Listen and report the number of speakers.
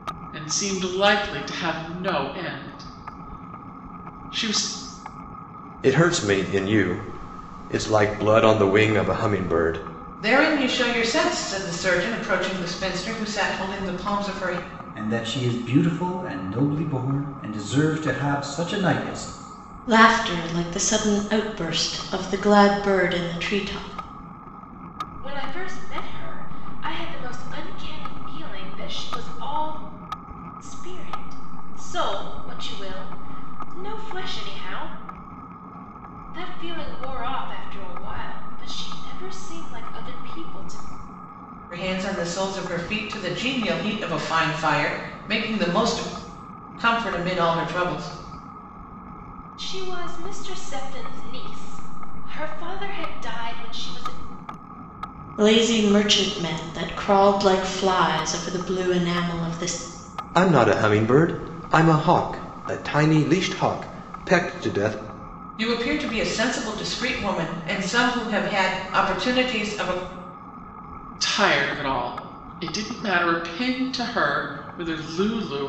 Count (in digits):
6